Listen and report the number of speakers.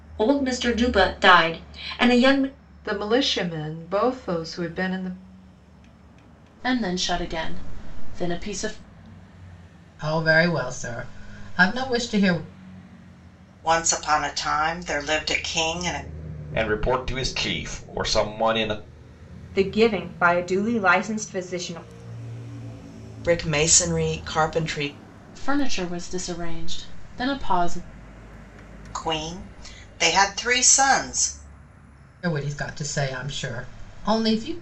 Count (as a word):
eight